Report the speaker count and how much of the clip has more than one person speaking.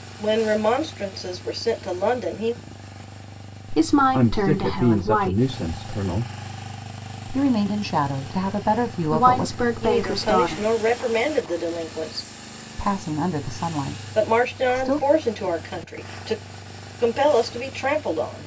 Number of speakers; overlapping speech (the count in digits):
4, about 21%